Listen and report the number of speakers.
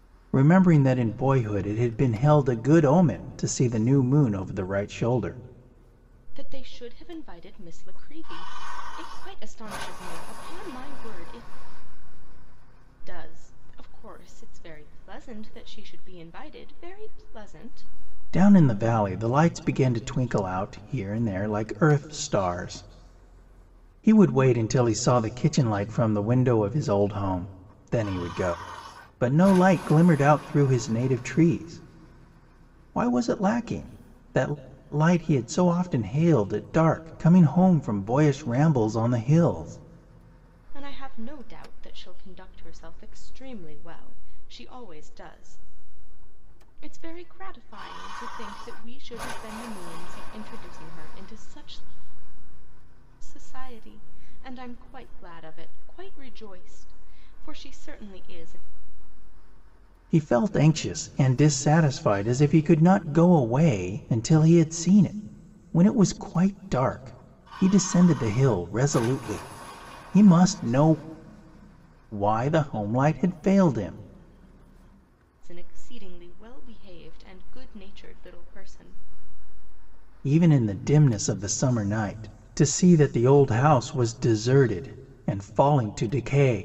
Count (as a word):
two